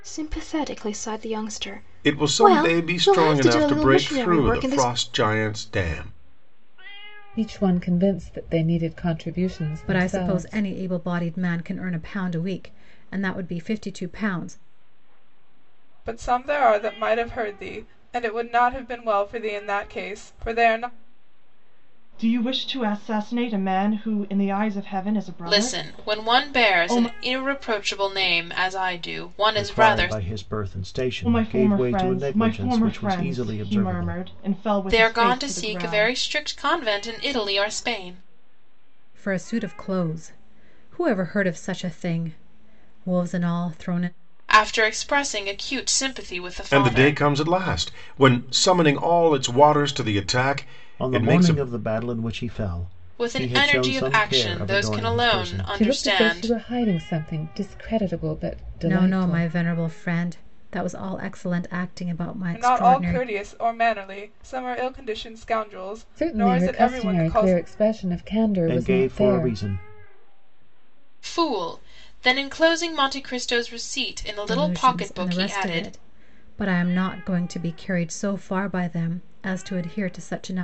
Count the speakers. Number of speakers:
8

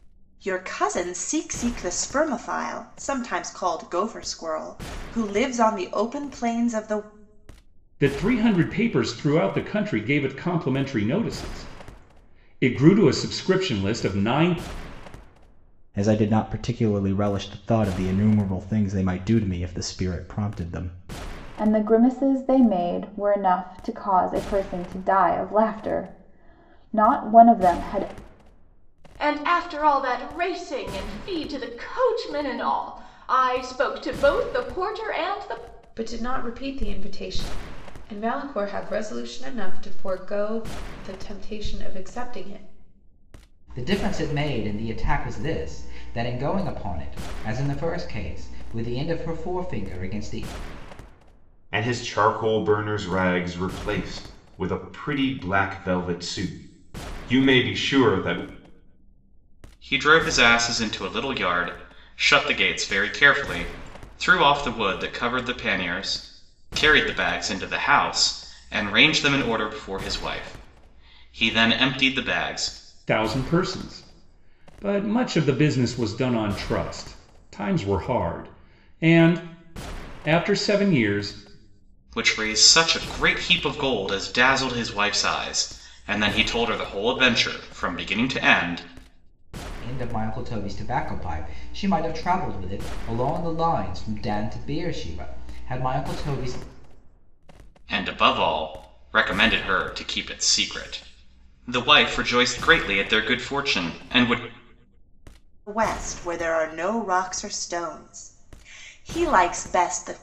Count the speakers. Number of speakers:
9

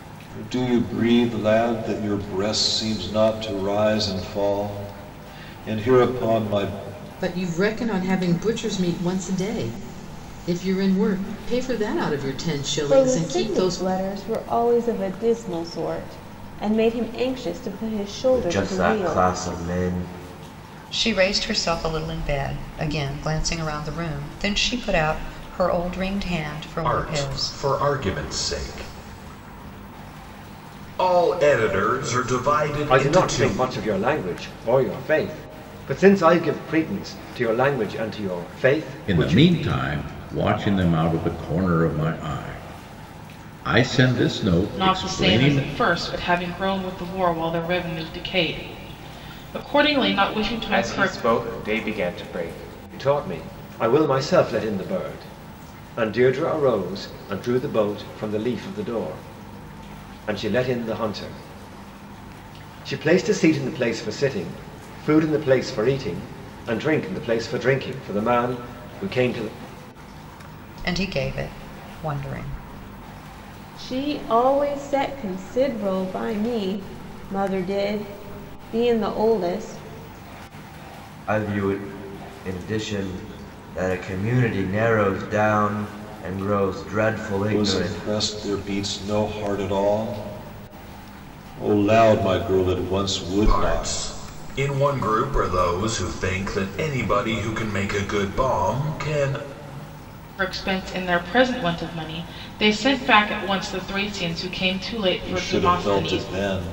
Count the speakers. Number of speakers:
10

